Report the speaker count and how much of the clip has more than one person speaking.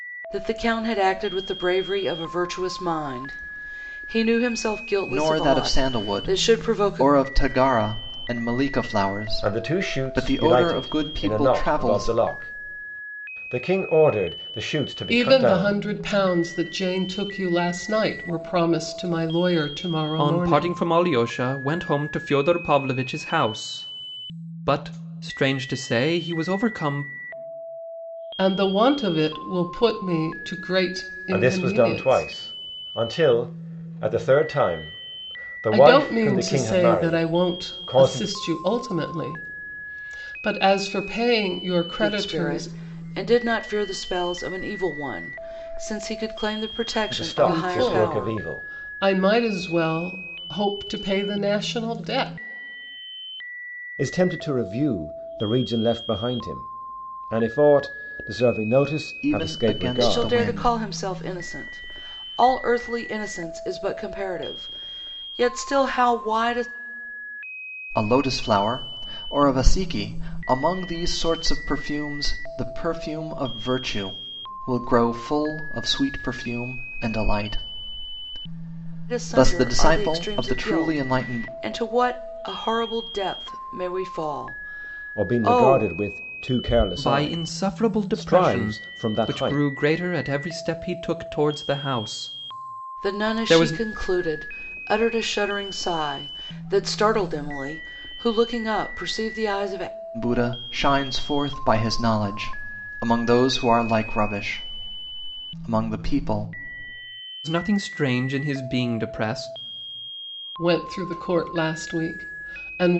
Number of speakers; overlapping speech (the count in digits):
5, about 18%